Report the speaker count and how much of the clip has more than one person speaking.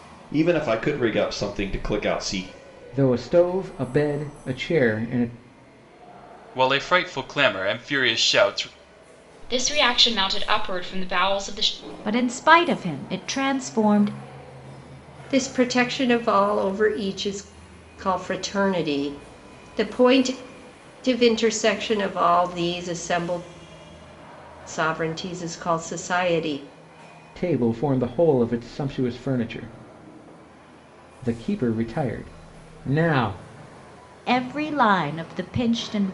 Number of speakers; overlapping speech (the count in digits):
6, no overlap